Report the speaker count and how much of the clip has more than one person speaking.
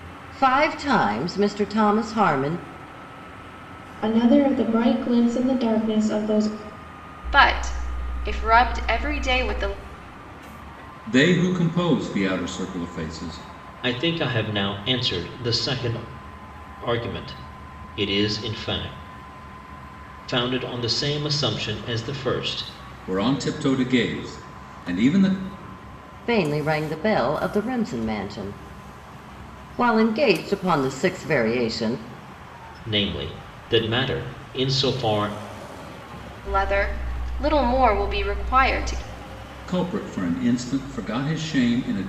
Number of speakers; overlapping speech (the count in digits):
5, no overlap